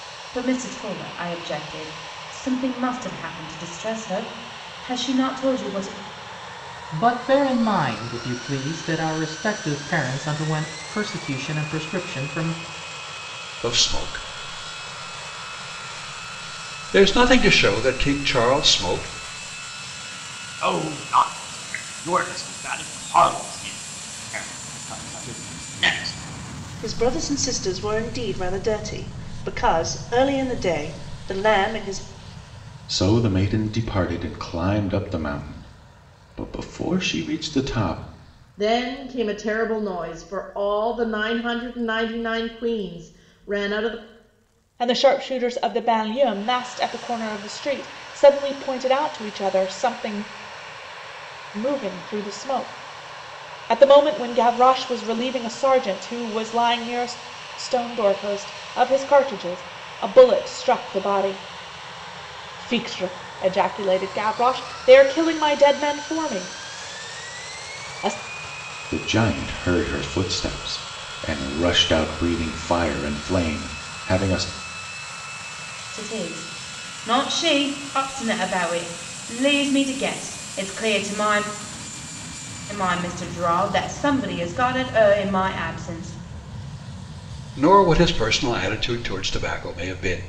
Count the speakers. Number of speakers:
8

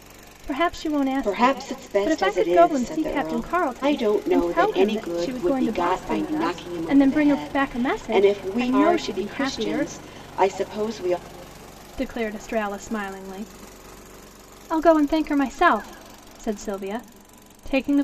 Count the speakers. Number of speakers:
2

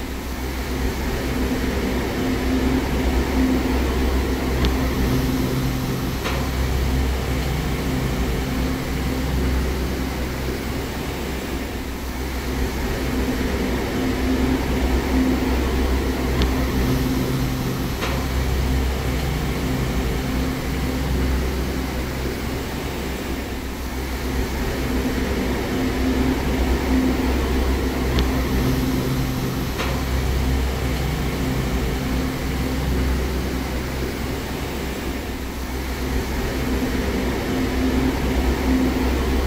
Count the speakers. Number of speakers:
0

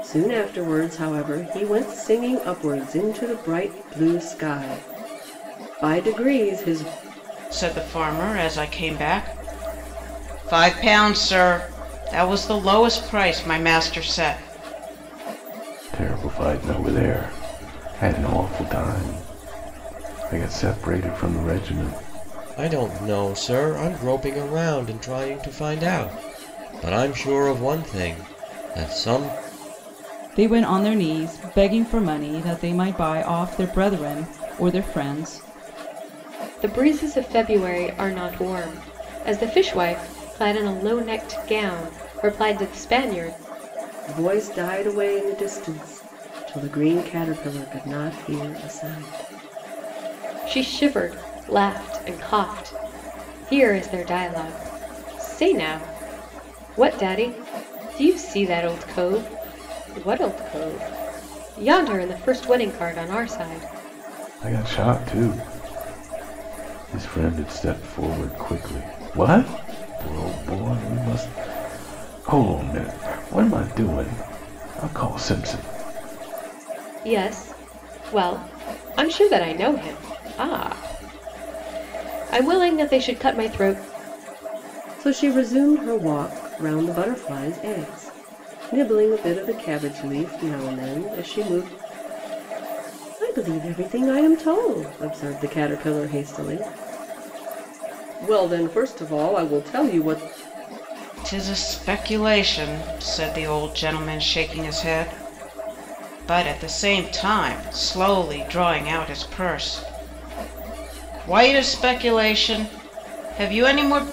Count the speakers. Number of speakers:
6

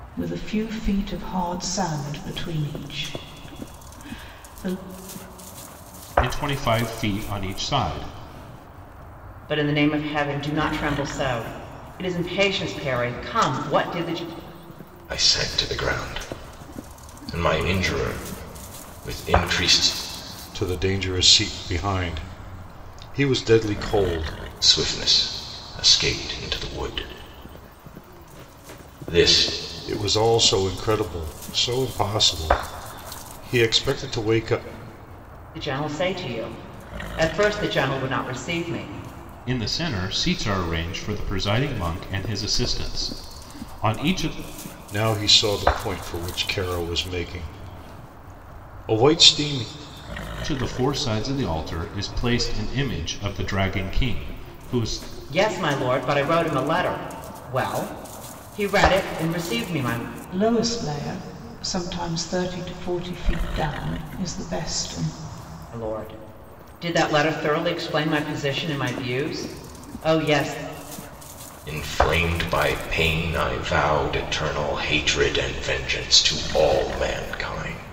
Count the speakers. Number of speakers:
5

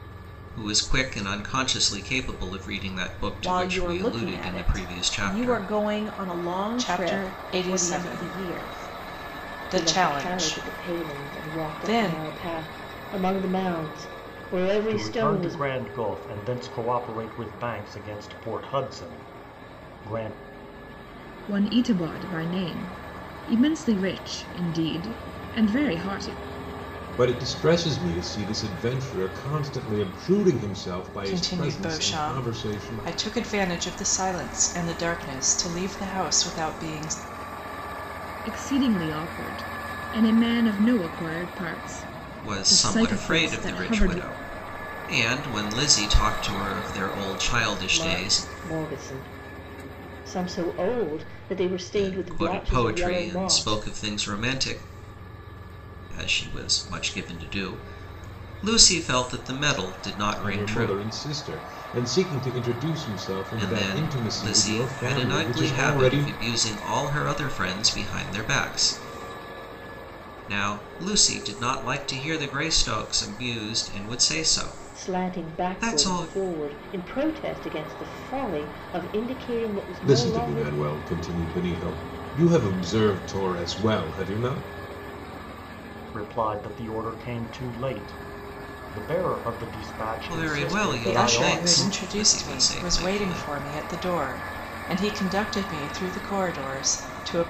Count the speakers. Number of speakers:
7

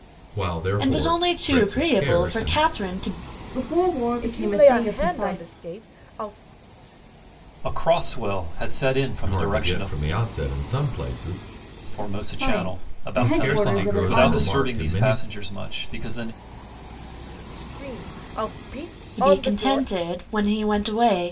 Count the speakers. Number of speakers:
5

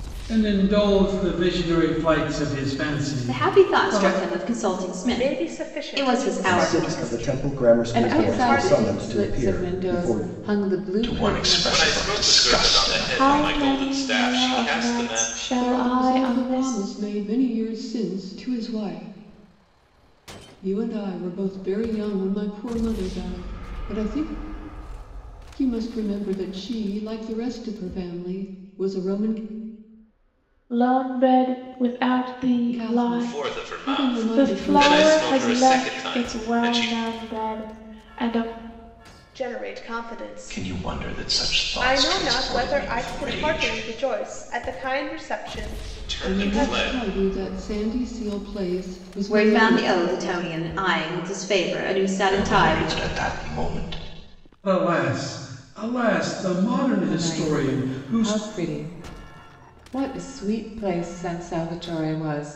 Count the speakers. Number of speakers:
9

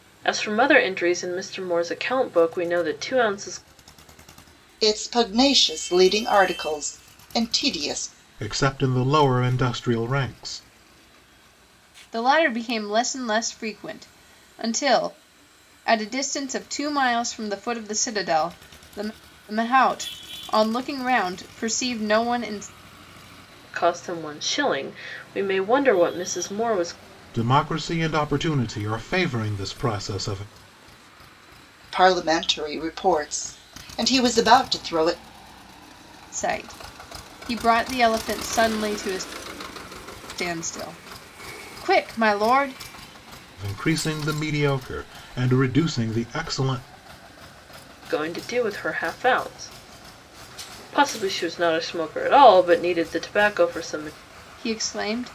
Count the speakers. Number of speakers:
4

